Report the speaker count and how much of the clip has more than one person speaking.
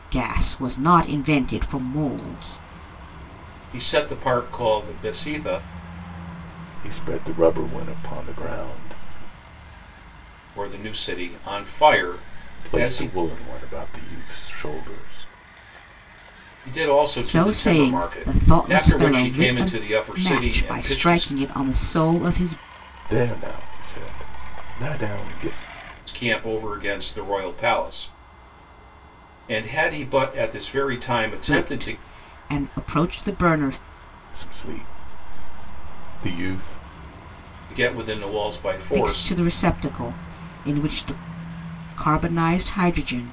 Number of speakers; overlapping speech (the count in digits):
3, about 12%